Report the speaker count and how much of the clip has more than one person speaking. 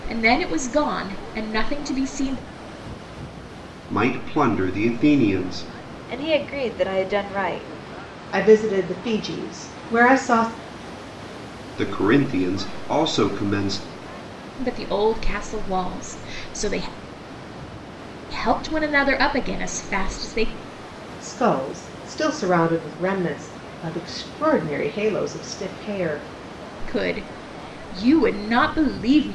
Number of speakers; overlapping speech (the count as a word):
four, no overlap